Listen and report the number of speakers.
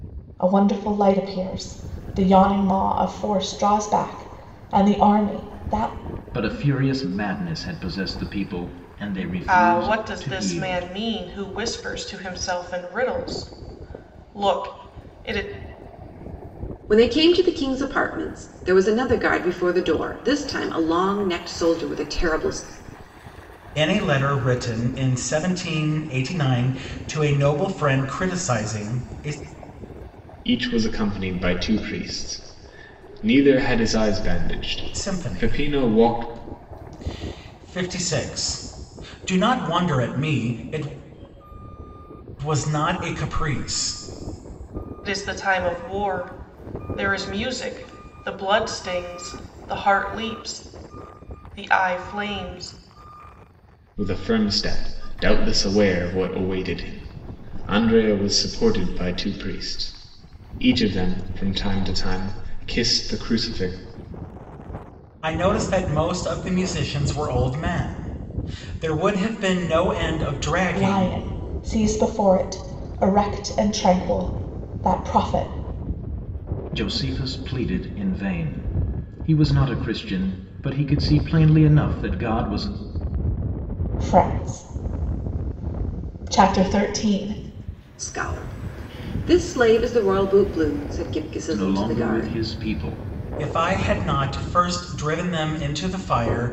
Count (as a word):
six